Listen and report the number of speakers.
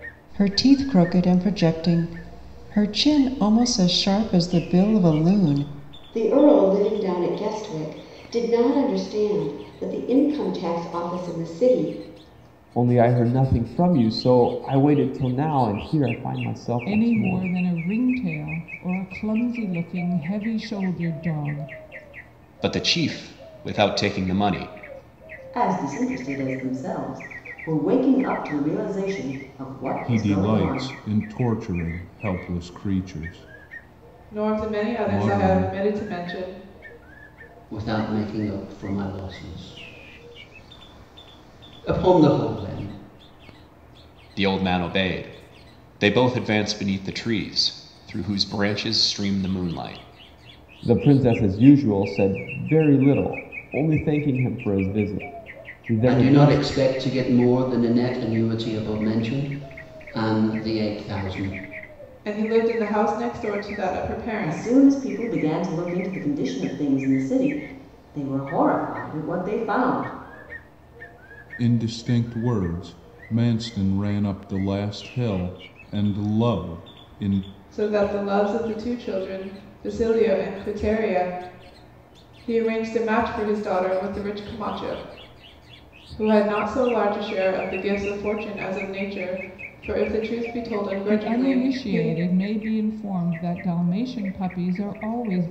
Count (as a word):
nine